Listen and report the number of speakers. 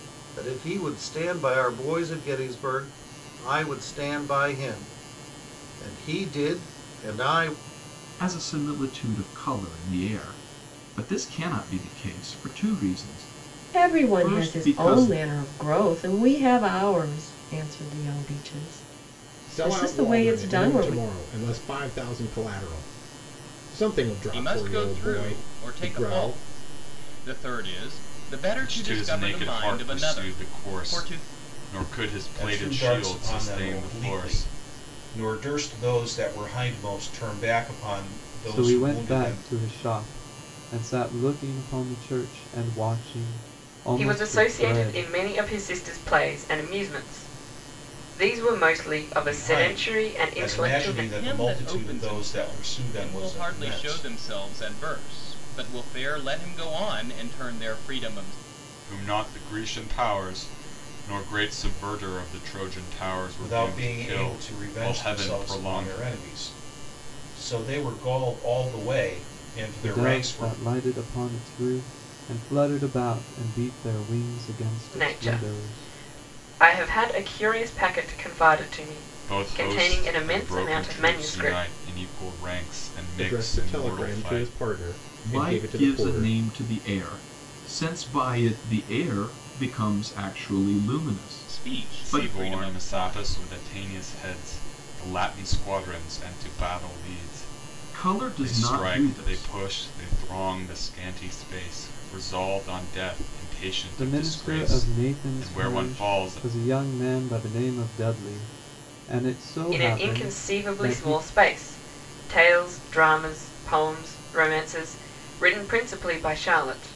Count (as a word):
nine